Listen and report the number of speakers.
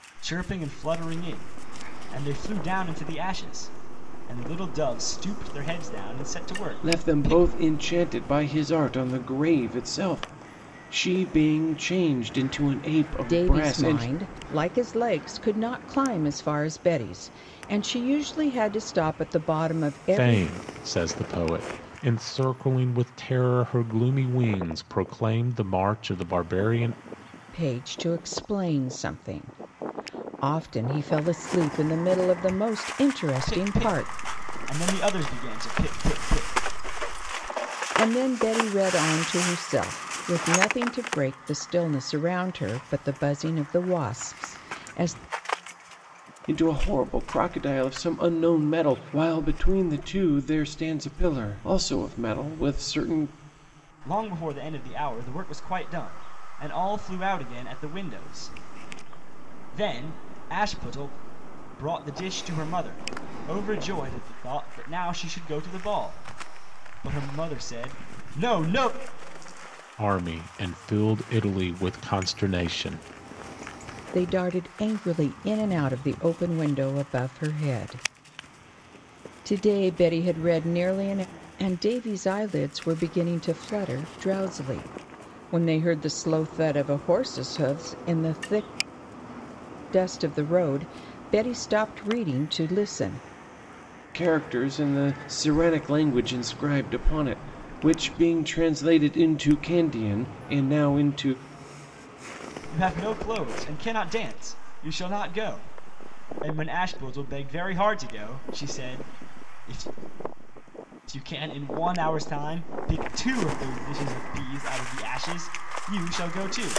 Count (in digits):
4